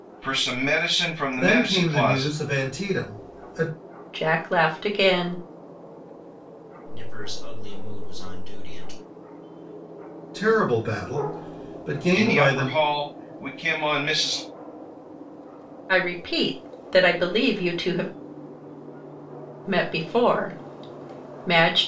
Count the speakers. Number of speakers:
4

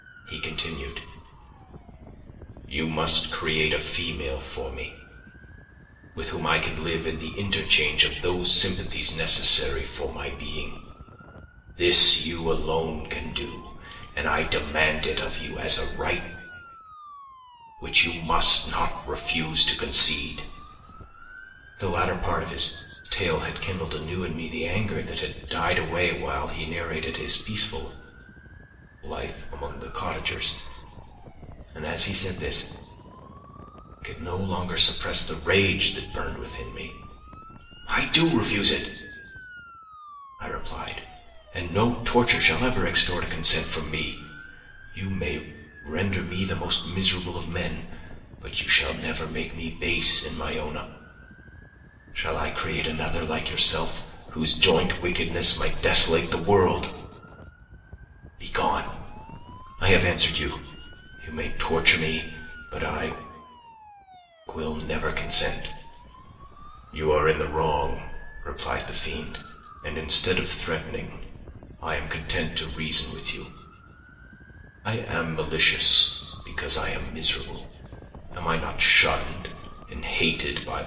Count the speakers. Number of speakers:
1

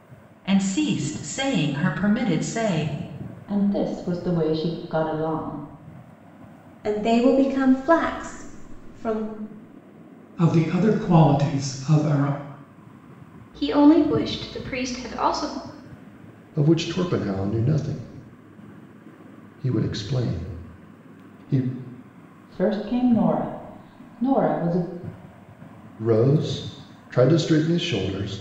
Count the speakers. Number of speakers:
6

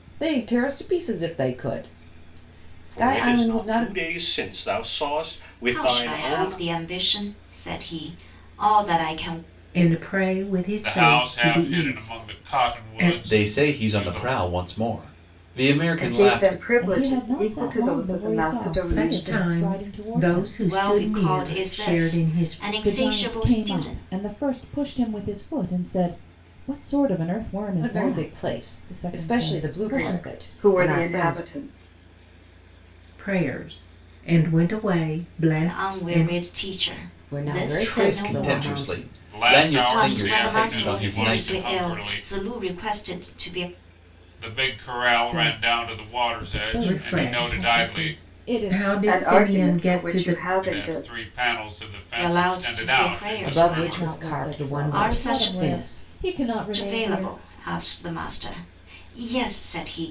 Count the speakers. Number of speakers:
8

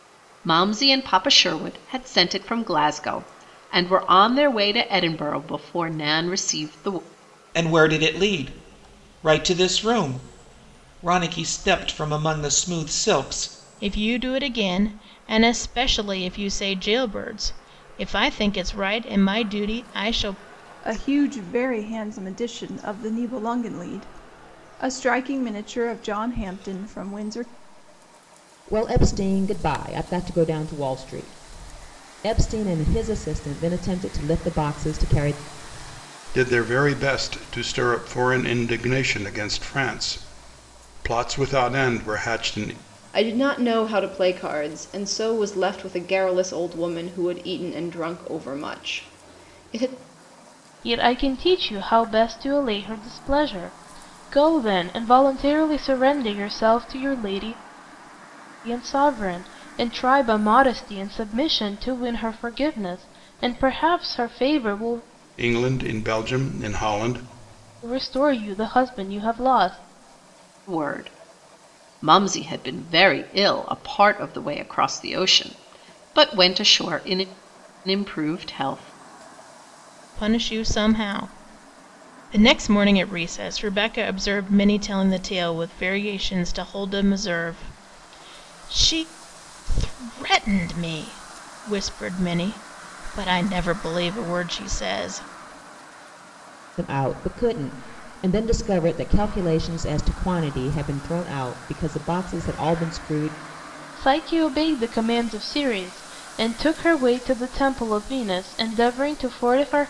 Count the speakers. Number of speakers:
8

